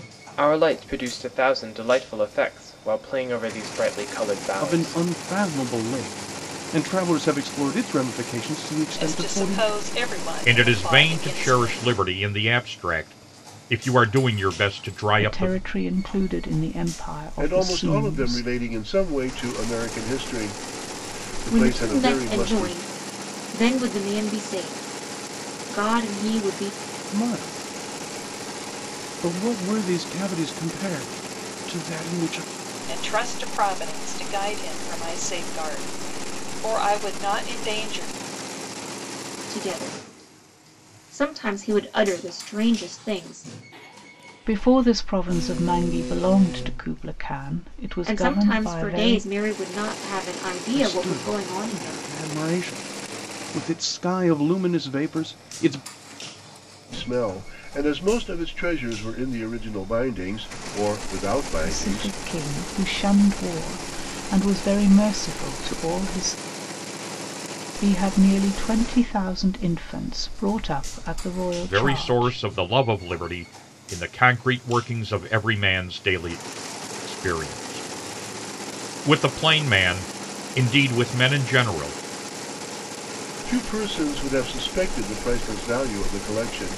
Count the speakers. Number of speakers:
seven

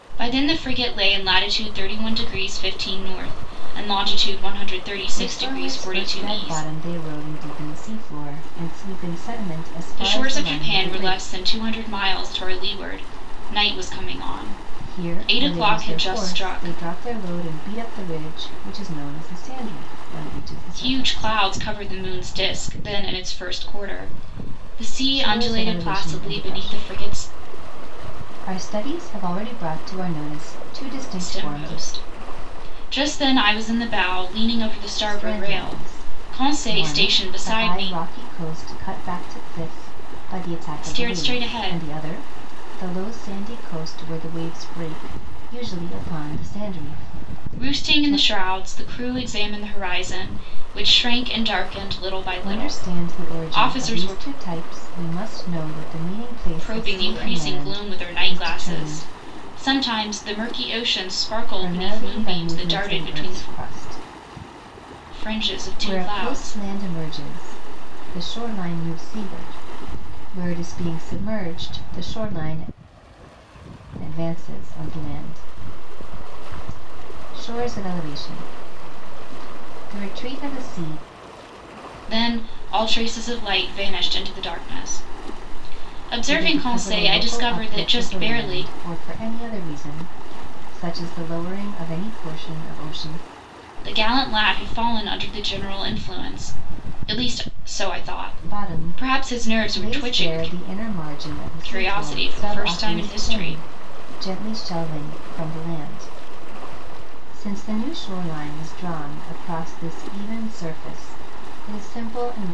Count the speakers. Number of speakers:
two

